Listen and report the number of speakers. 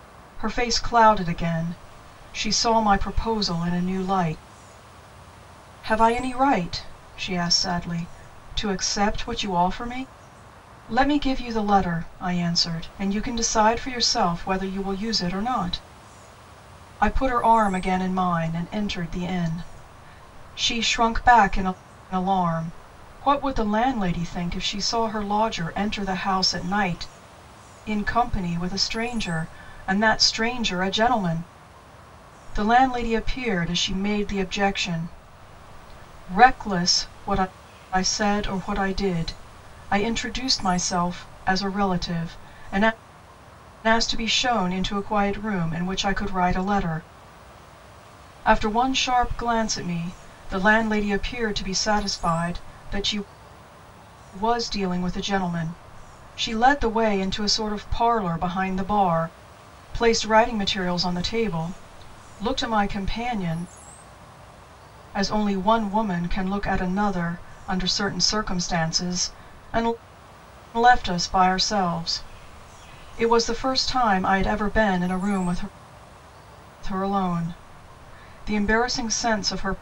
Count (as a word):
one